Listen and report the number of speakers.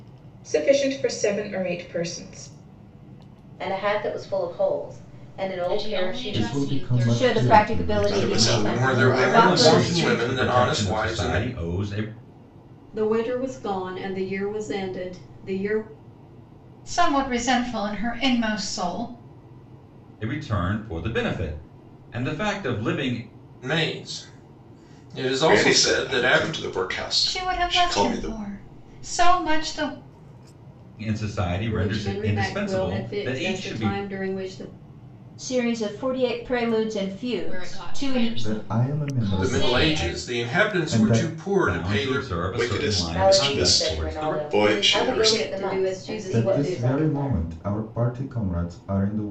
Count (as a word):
ten